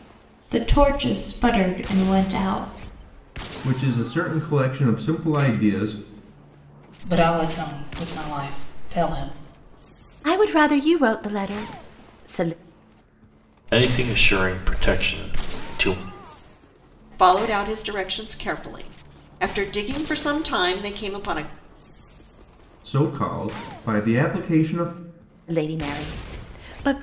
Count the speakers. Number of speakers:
6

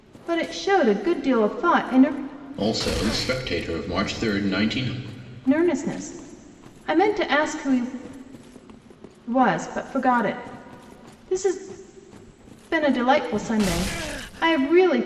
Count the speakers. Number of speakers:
2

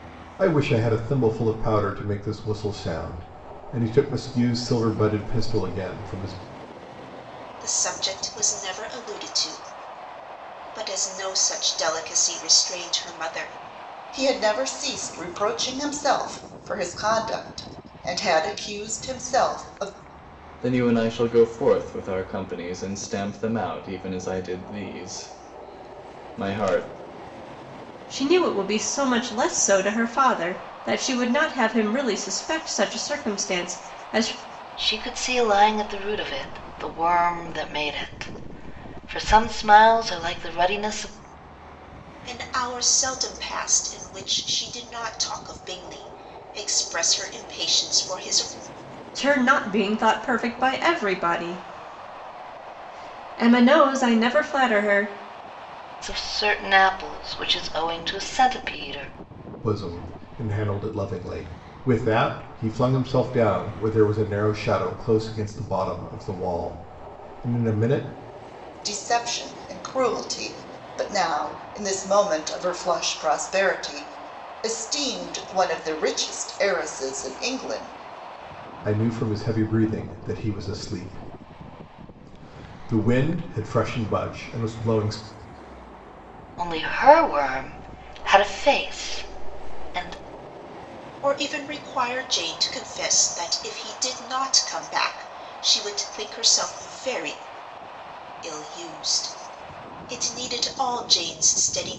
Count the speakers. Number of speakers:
6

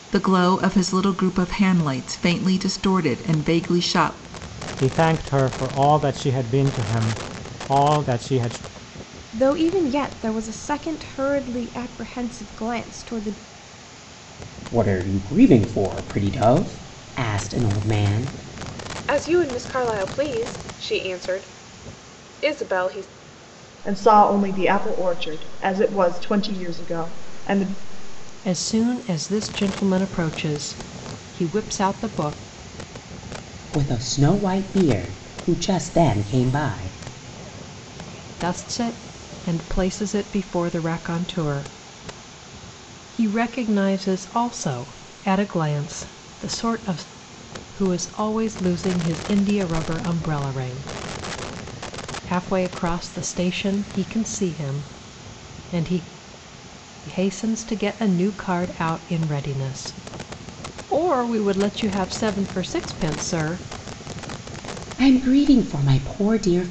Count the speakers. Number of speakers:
7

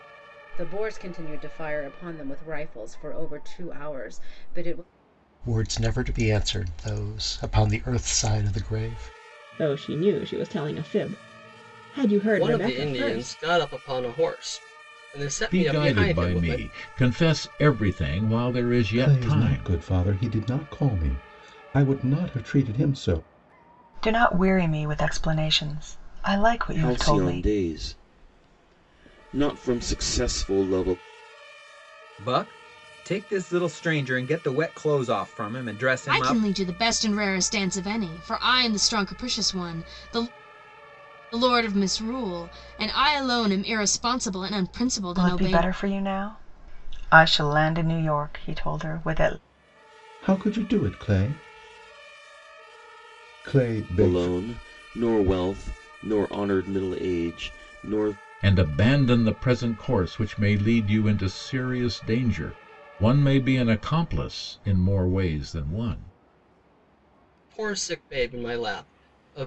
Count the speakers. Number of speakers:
10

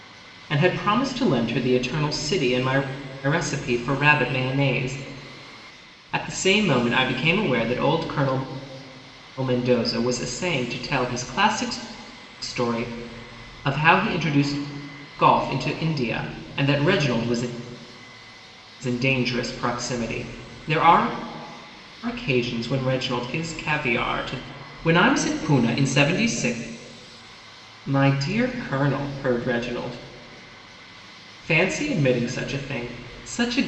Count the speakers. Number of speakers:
1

